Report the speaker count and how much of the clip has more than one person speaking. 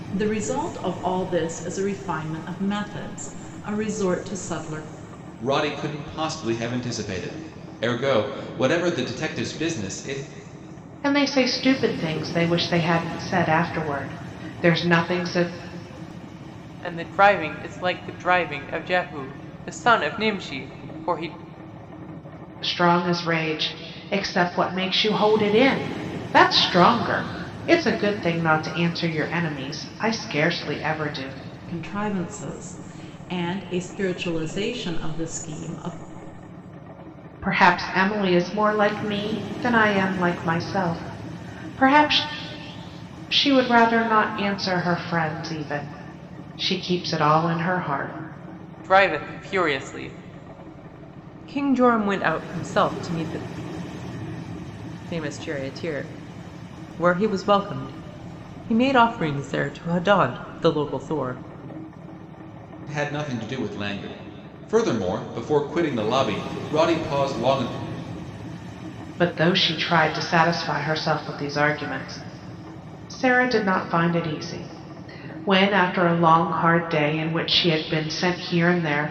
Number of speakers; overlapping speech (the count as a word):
four, no overlap